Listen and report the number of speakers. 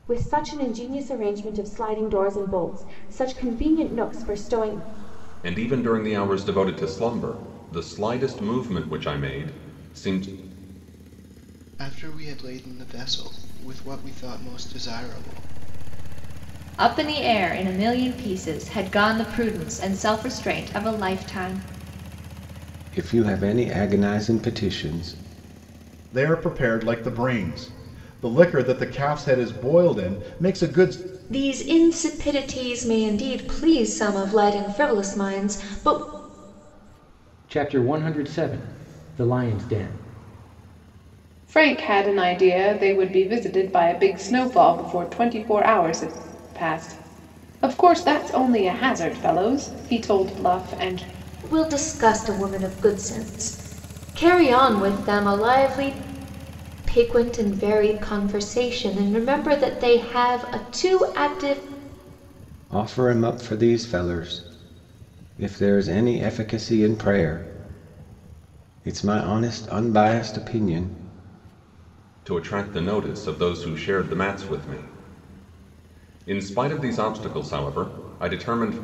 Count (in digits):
9